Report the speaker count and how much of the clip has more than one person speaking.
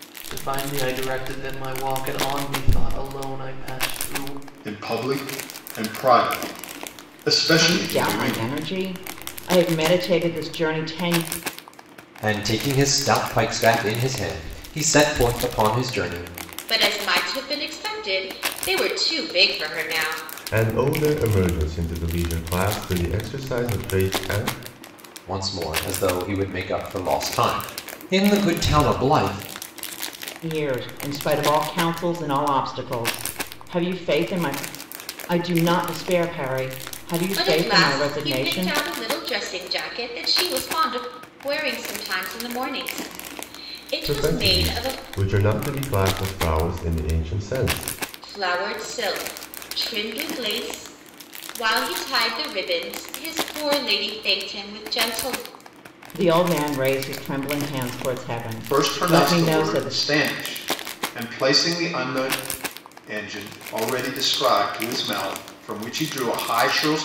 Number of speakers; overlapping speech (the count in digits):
6, about 8%